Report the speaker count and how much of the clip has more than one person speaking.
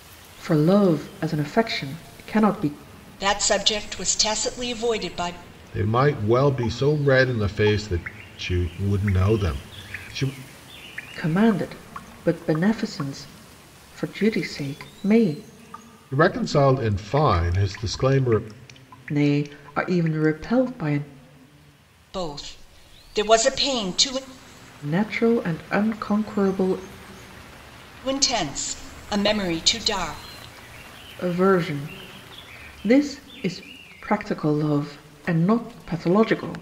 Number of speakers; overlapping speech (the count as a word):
three, no overlap